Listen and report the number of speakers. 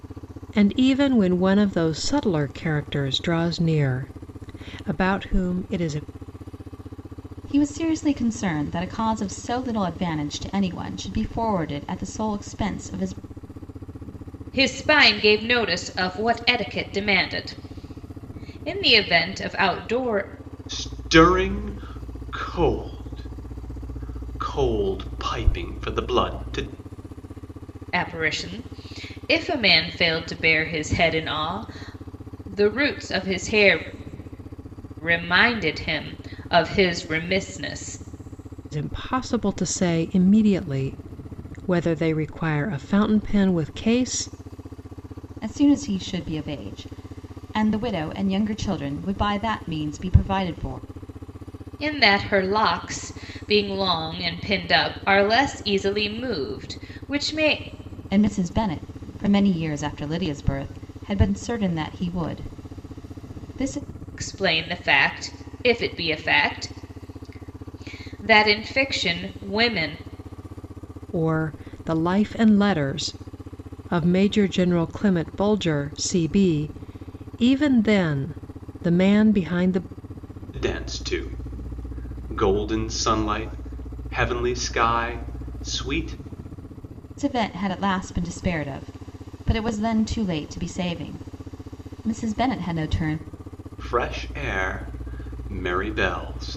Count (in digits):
4